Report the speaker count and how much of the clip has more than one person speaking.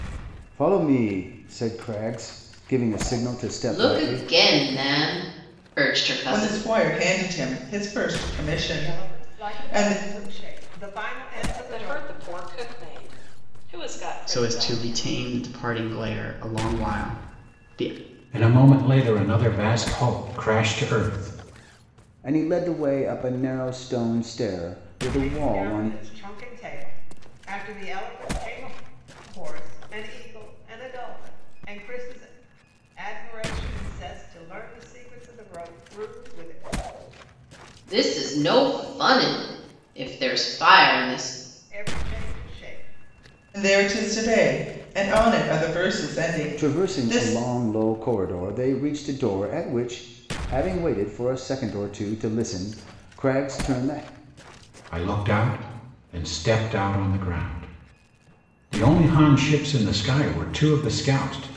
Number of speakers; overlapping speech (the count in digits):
7, about 9%